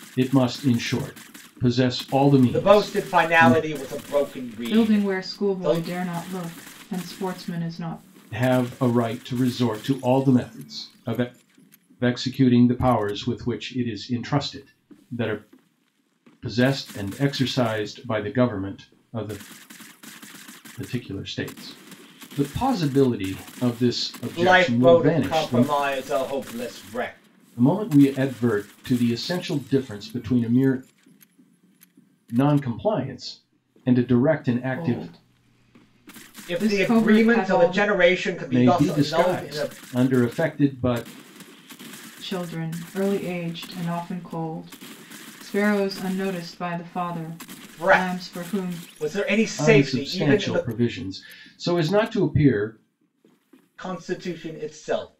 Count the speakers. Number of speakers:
3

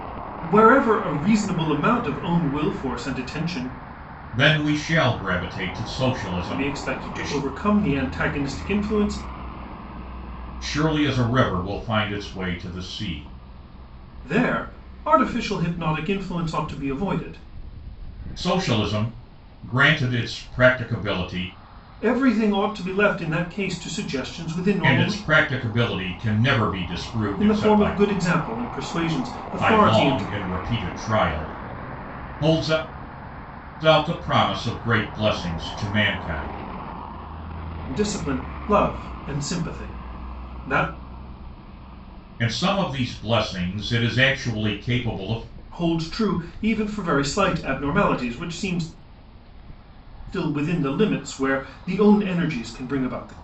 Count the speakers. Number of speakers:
2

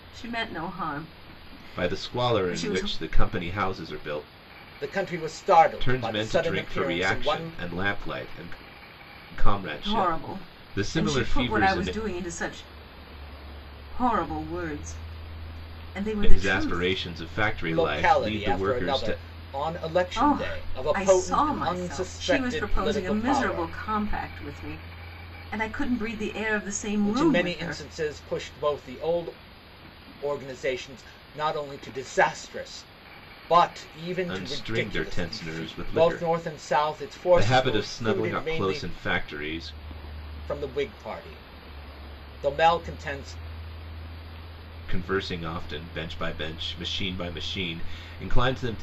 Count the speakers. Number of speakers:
3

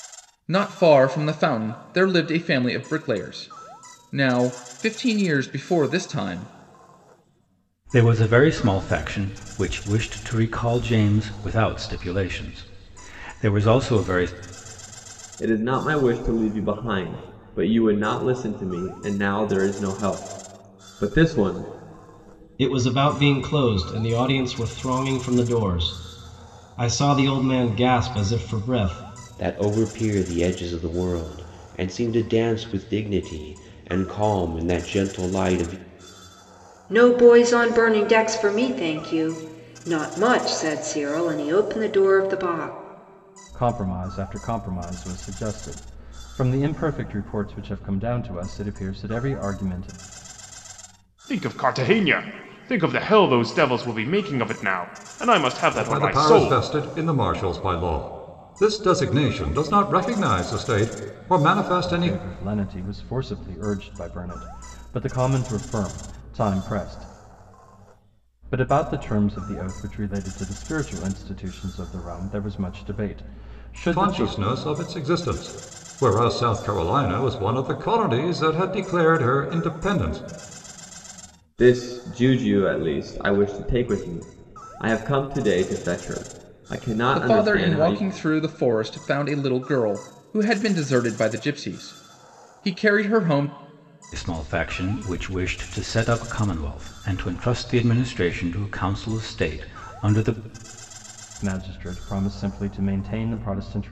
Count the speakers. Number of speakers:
9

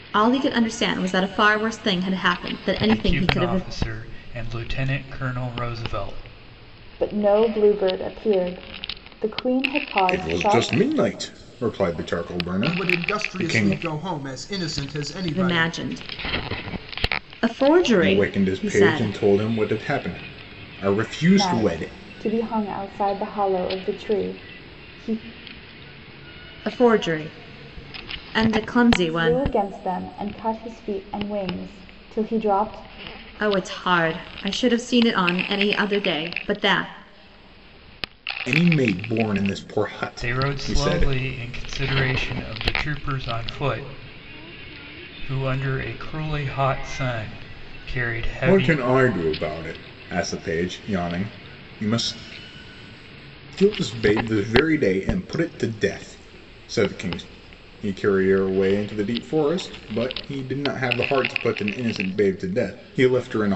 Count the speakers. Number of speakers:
5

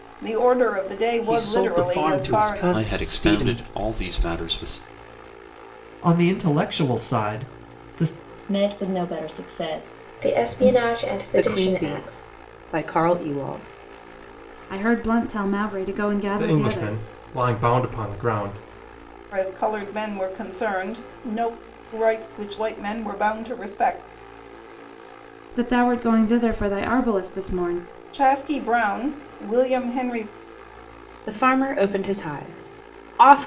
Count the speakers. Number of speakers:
9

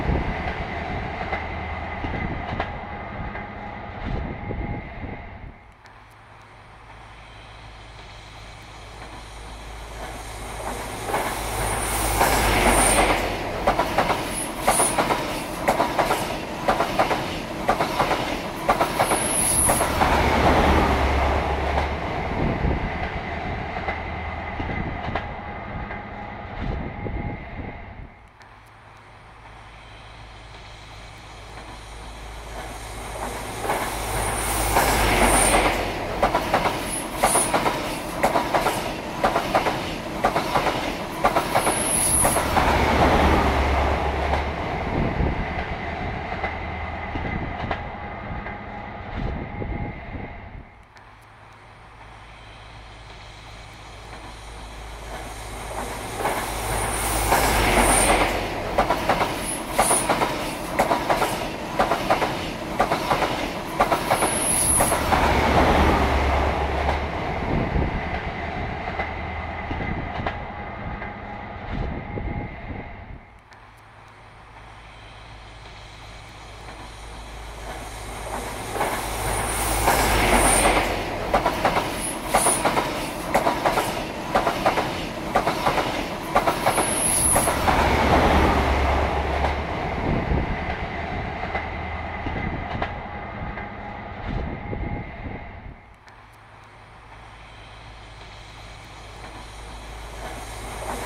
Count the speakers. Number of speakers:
0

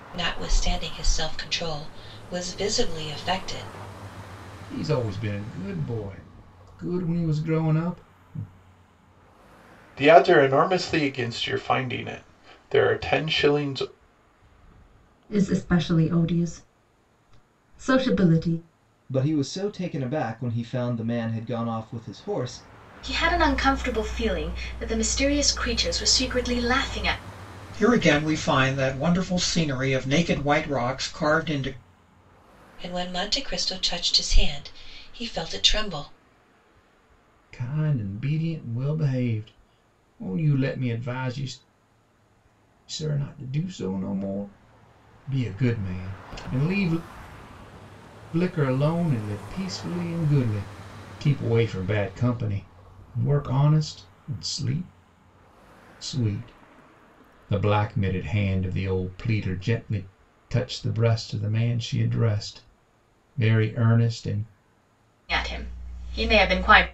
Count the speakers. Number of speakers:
7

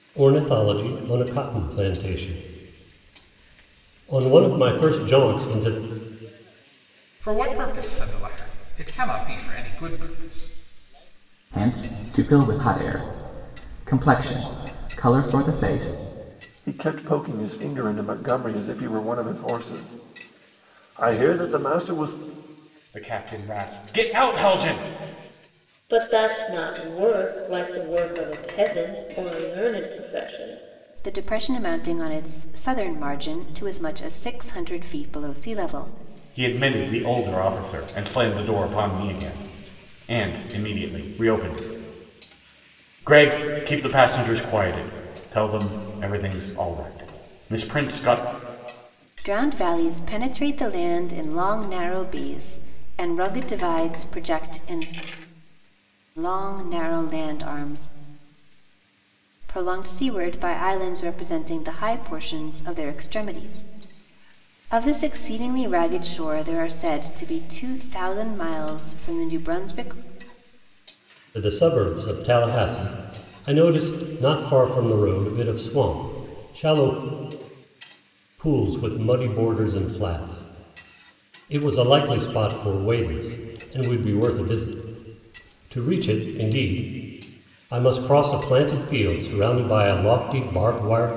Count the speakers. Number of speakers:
7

